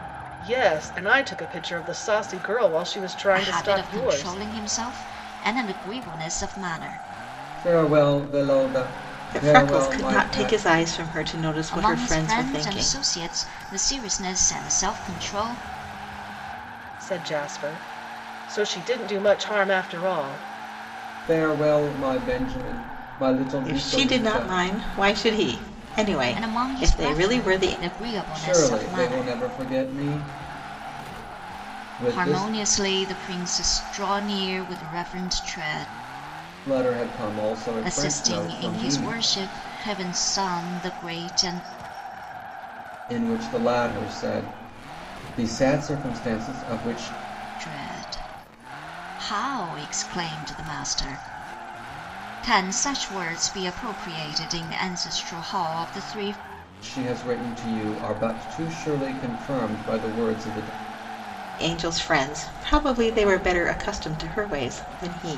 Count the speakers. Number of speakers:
4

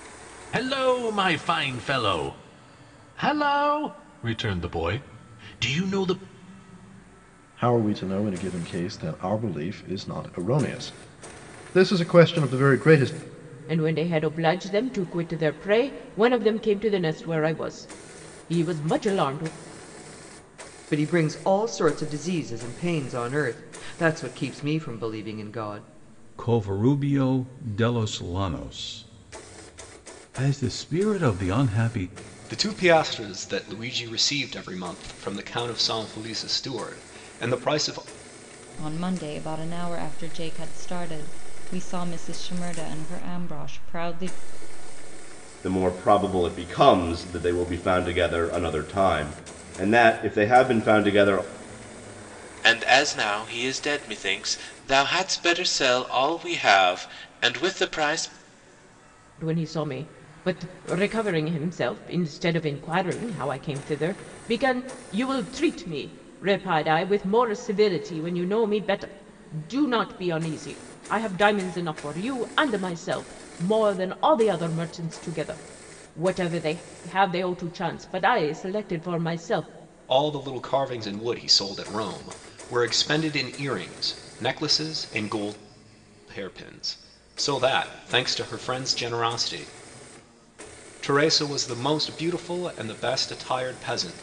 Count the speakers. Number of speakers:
9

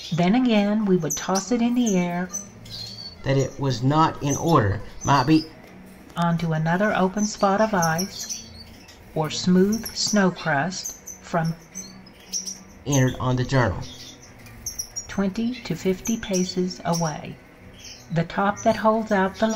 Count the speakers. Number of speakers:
2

